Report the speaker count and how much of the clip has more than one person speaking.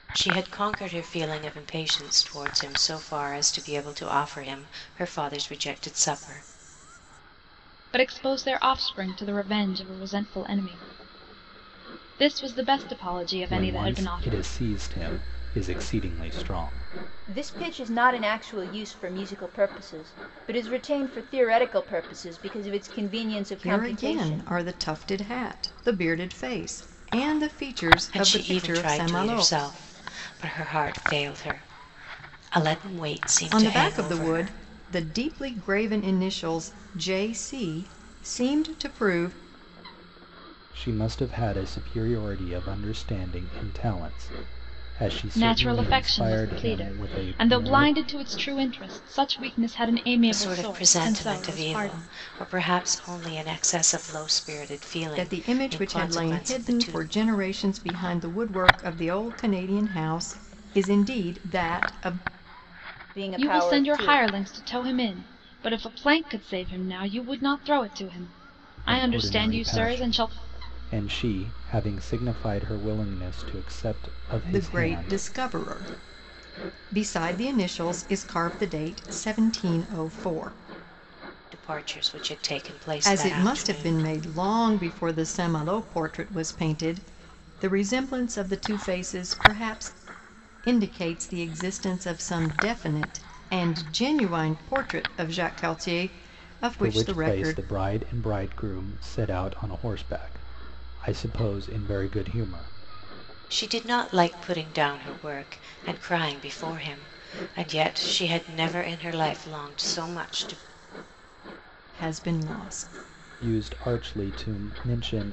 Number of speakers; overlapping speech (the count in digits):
5, about 14%